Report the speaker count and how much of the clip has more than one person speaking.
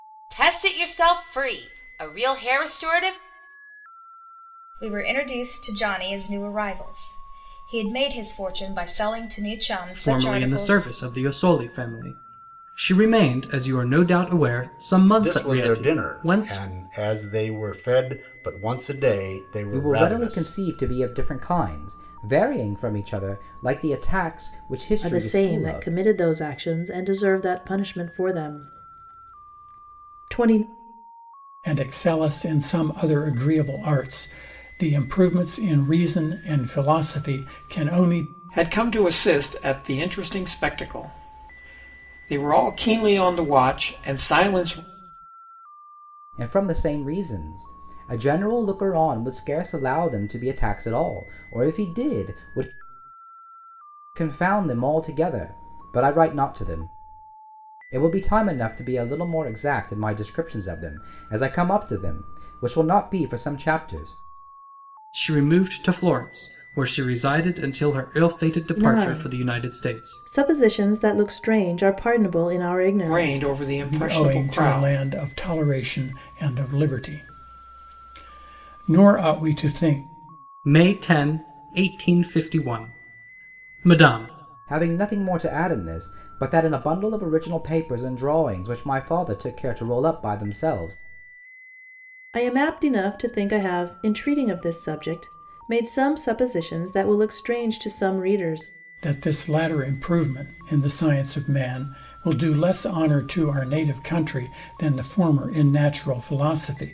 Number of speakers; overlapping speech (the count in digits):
8, about 7%